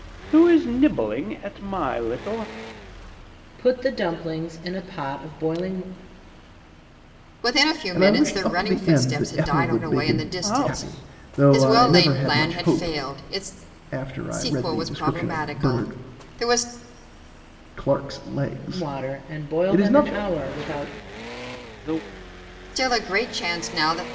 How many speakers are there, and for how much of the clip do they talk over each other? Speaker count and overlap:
4, about 35%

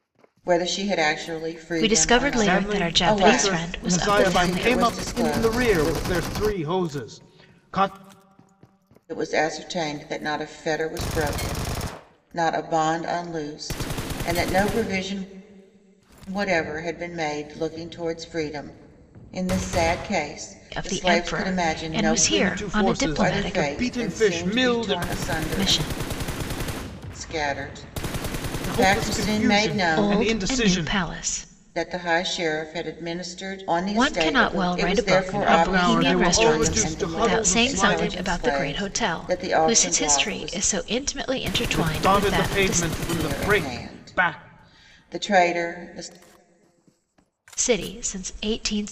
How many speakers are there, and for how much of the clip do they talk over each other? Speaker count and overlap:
3, about 42%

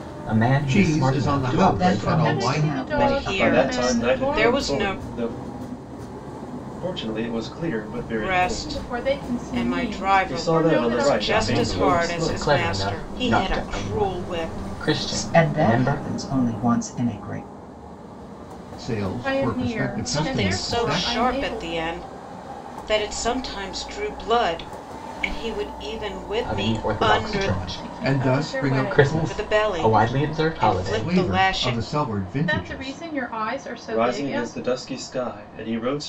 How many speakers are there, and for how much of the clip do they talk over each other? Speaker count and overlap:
6, about 59%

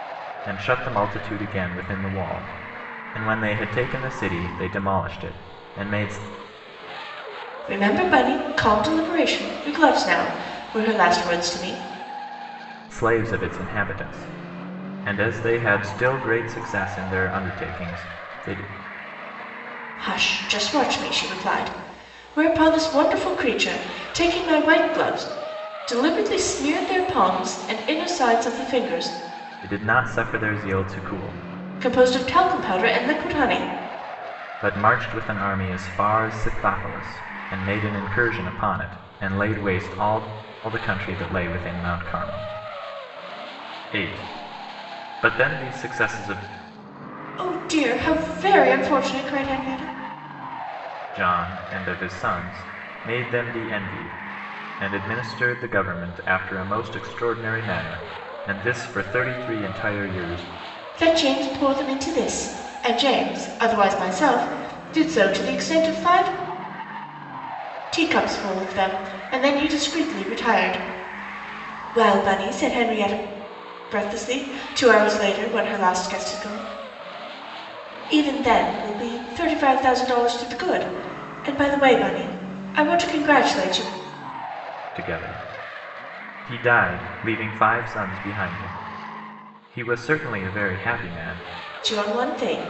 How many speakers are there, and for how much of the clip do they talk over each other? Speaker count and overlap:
2, no overlap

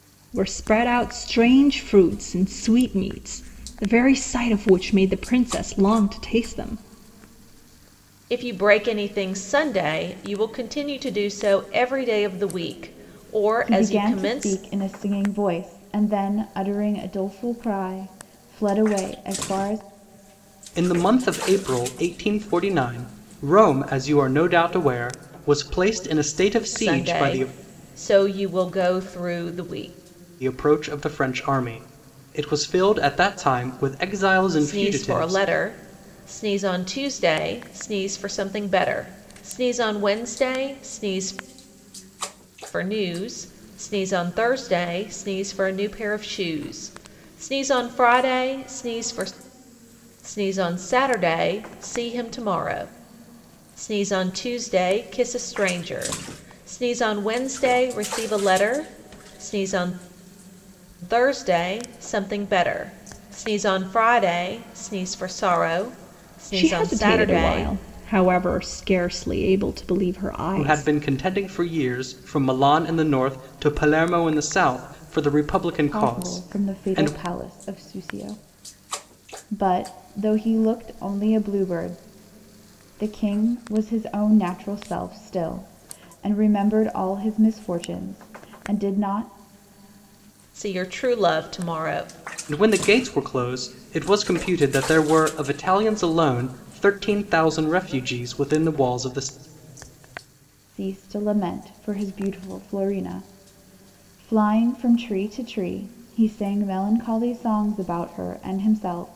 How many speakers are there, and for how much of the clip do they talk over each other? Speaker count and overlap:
4, about 5%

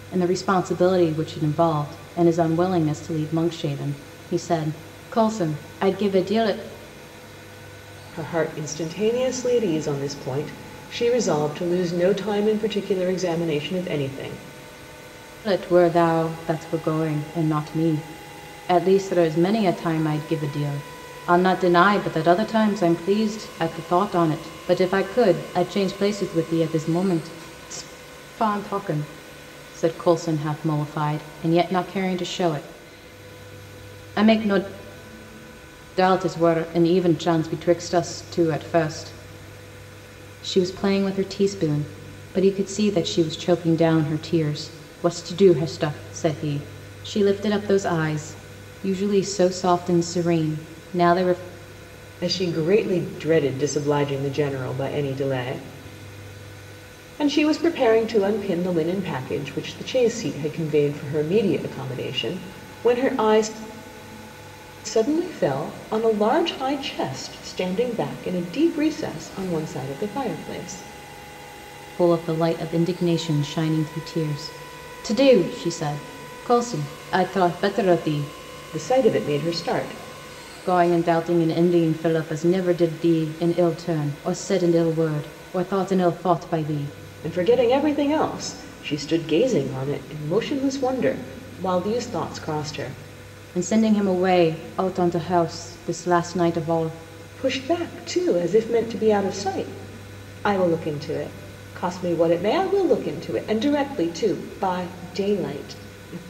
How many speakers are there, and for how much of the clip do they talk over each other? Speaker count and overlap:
2, no overlap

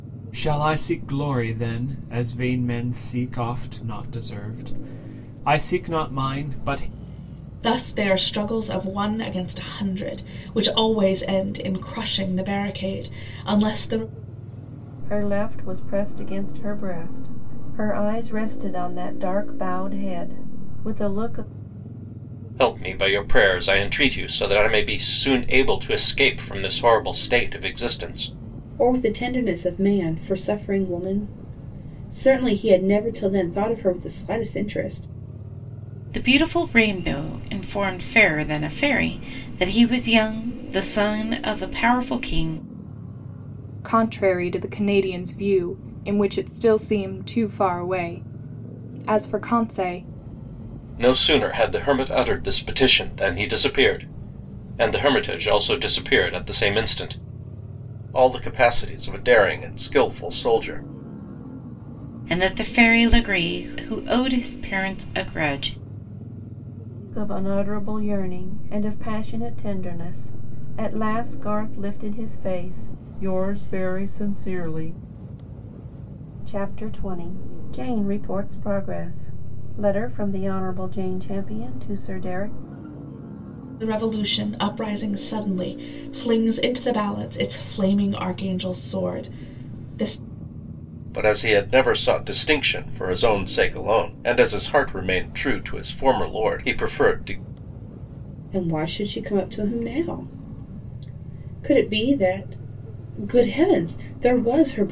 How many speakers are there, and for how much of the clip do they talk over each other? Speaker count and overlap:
7, no overlap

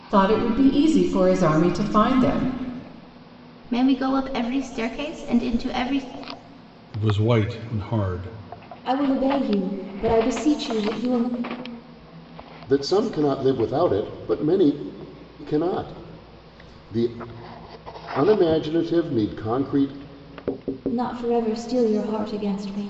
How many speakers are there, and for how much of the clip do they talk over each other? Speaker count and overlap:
5, no overlap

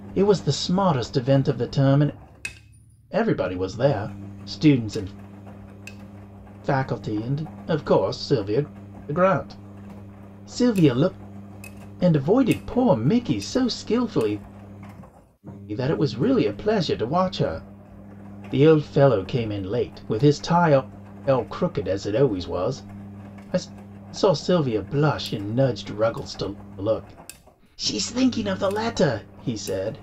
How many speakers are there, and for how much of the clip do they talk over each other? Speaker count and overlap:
1, no overlap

